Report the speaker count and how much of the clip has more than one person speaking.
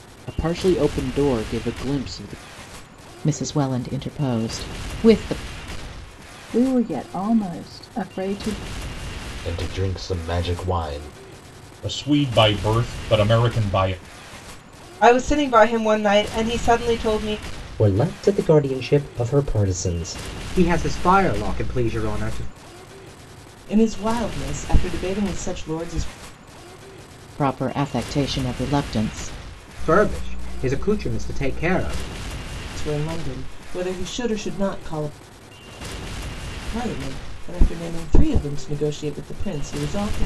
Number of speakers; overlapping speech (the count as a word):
nine, no overlap